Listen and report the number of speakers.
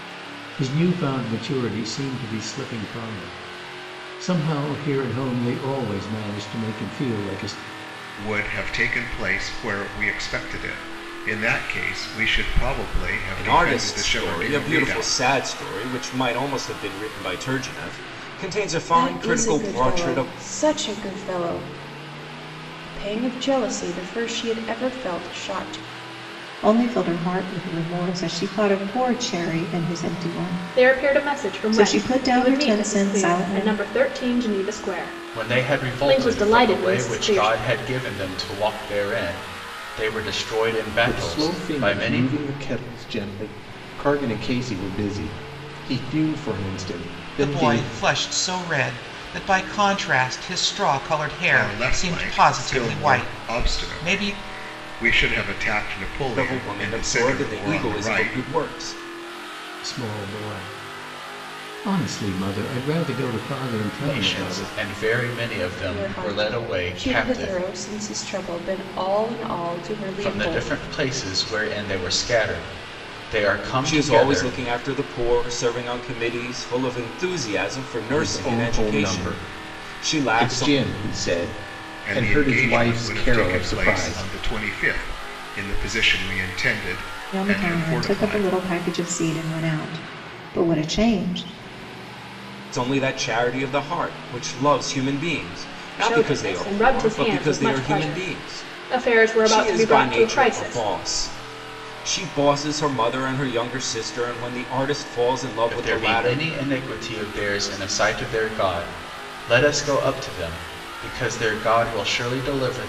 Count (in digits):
9